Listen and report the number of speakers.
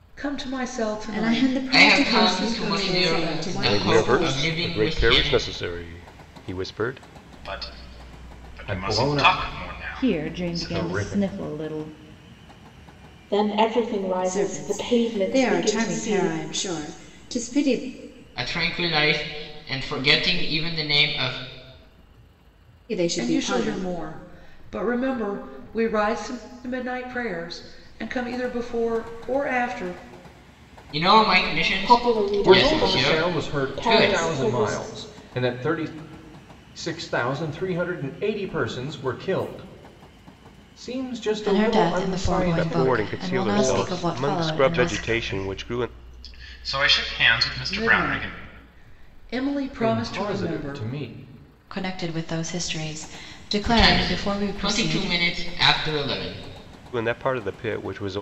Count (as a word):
eight